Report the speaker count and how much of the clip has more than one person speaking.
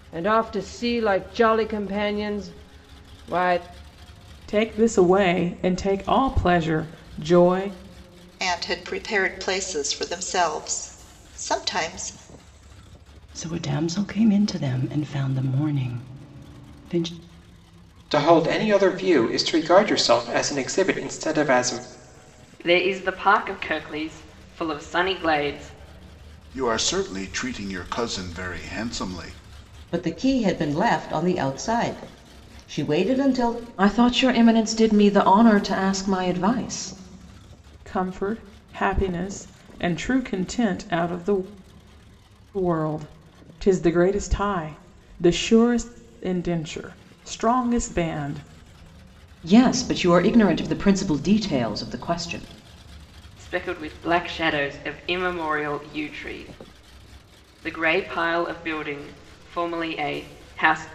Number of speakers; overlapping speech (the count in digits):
9, no overlap